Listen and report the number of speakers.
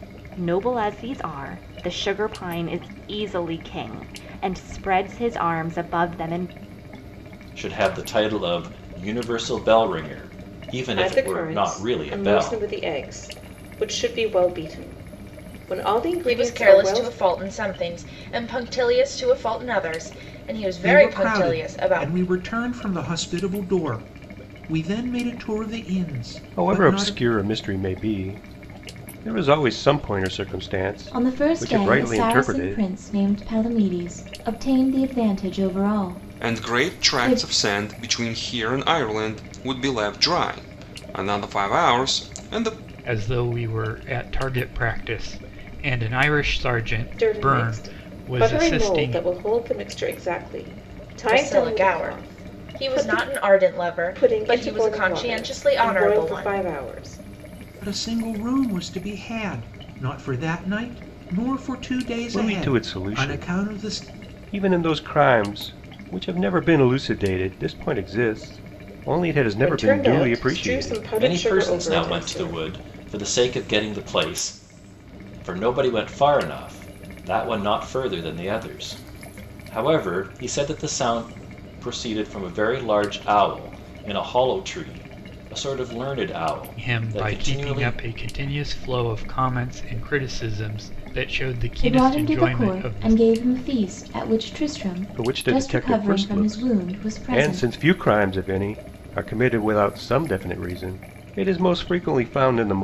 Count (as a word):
nine